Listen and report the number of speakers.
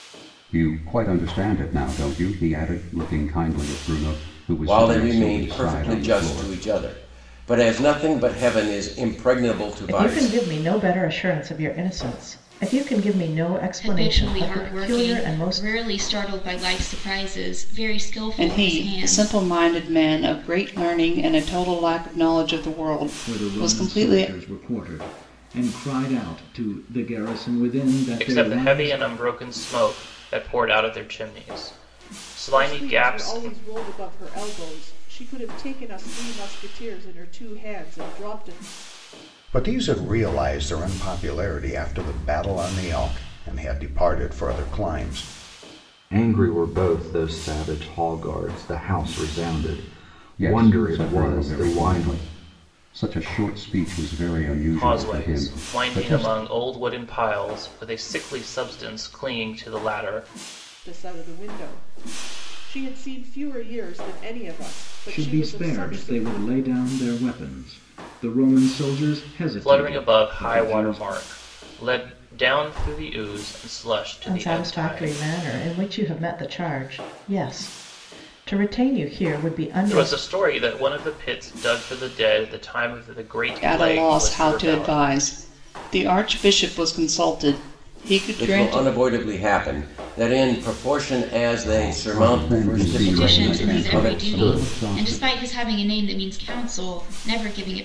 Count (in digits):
10